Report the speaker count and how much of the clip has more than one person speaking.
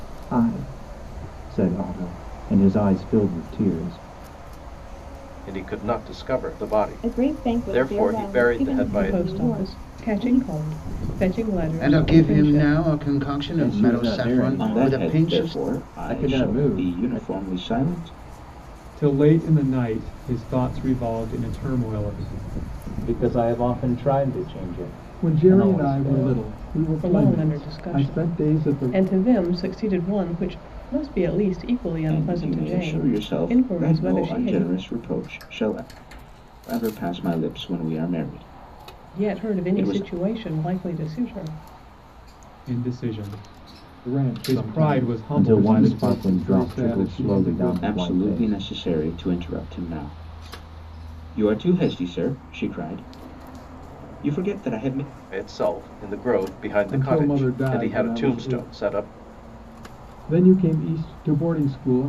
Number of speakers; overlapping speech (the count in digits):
10, about 36%